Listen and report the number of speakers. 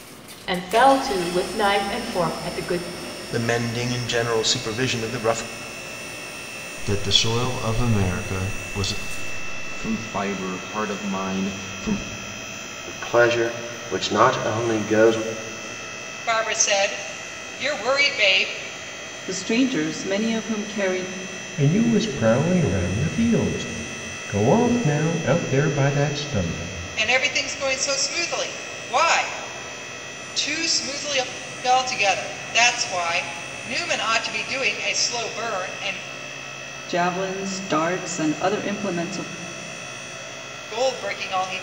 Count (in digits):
8